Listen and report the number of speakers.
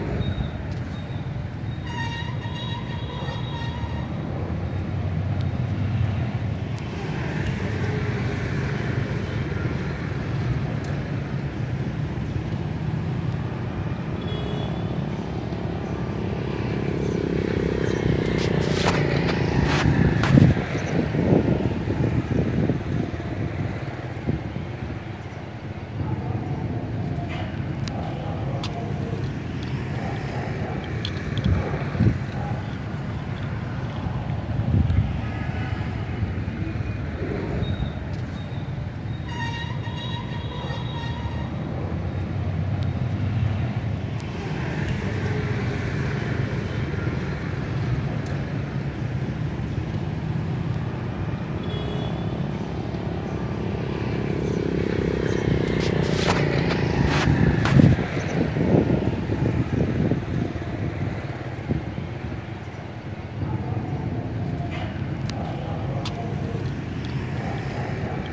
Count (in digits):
0